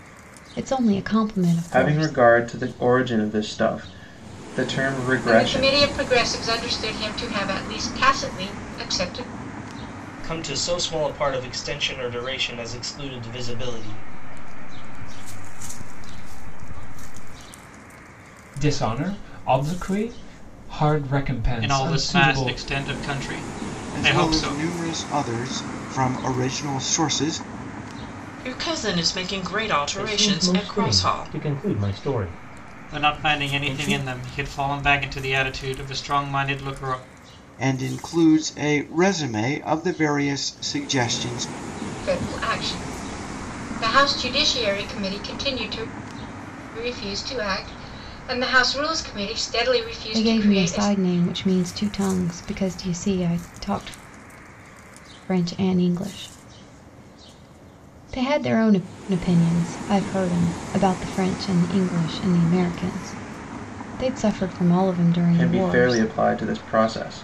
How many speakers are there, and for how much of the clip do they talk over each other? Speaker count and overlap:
ten, about 11%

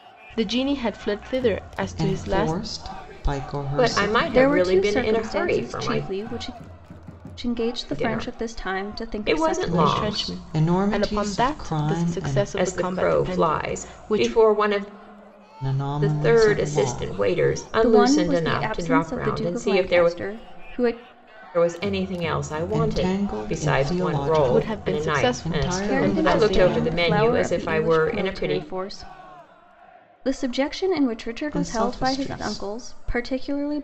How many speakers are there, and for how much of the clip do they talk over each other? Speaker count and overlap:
four, about 61%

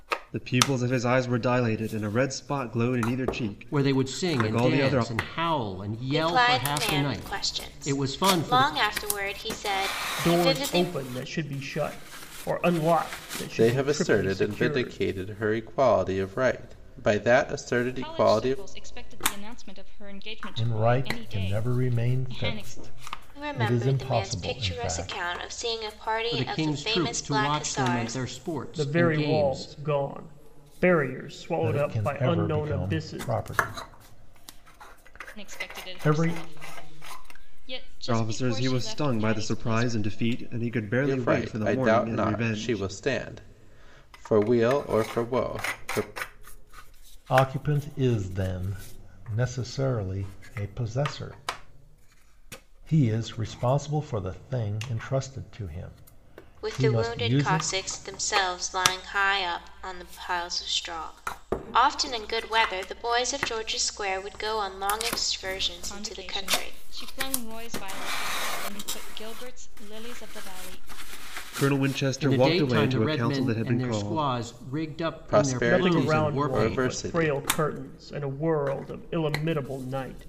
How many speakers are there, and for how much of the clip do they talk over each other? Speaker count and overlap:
seven, about 34%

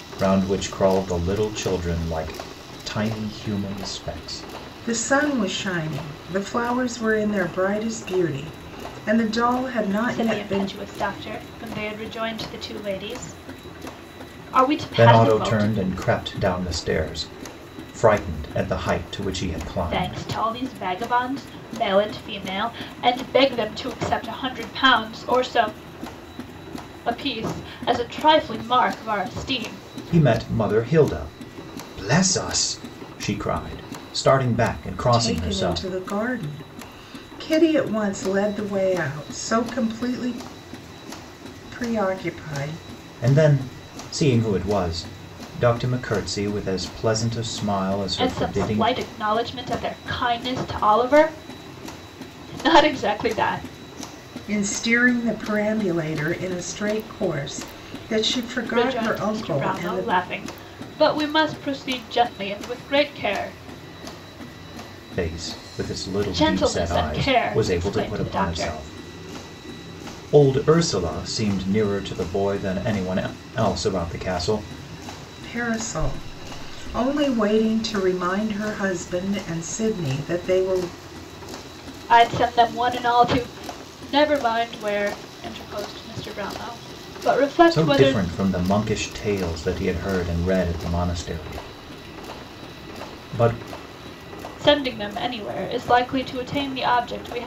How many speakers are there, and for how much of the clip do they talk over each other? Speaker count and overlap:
three, about 8%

